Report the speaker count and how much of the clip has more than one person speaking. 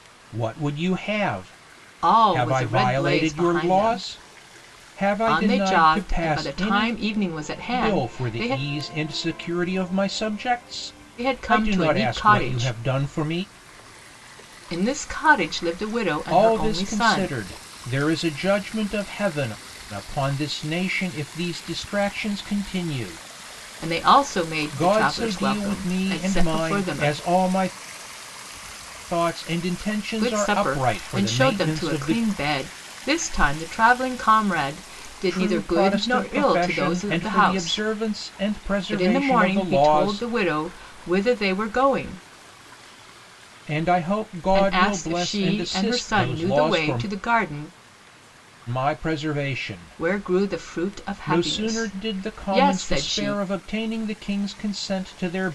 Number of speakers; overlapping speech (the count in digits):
2, about 39%